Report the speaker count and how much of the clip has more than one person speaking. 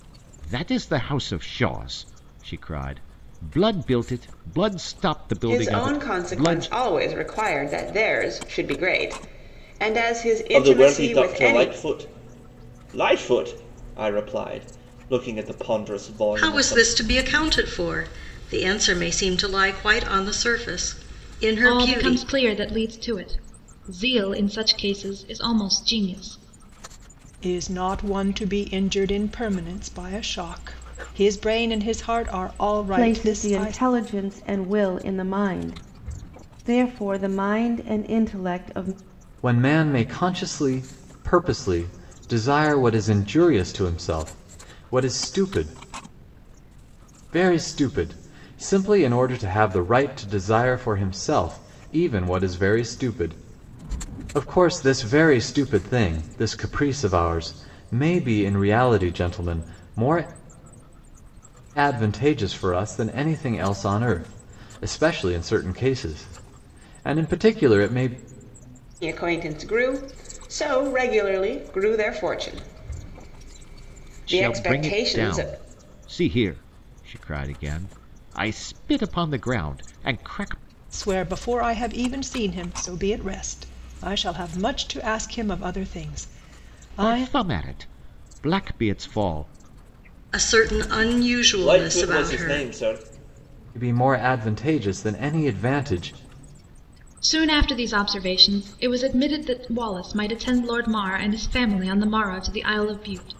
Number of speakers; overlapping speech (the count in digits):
8, about 7%